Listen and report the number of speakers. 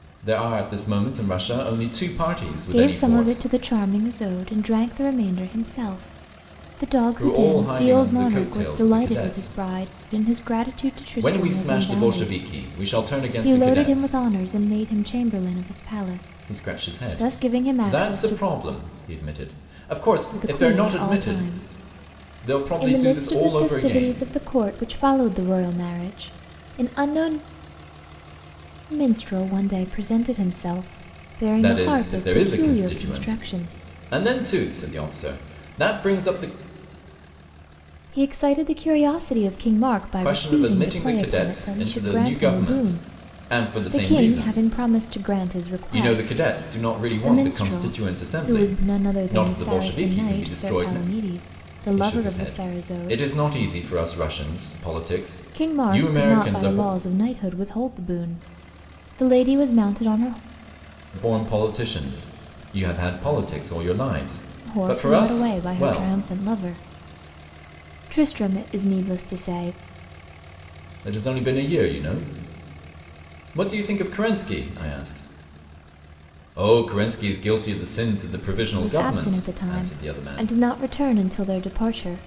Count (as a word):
two